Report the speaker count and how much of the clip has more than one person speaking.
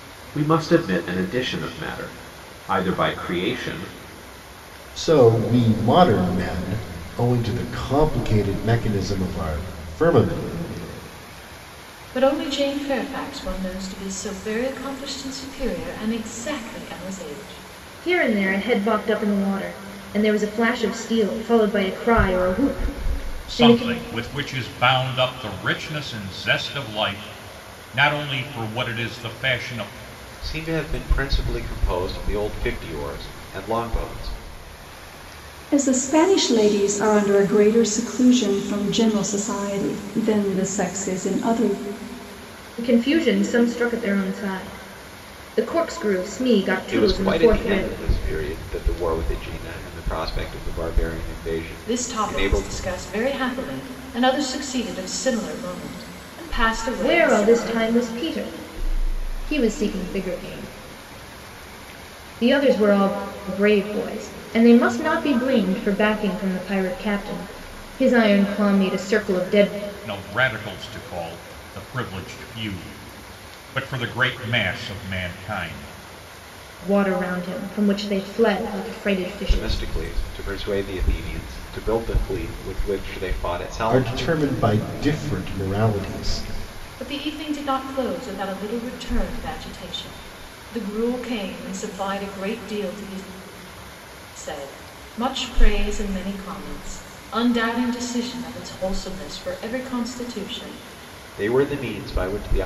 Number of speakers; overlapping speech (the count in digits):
7, about 4%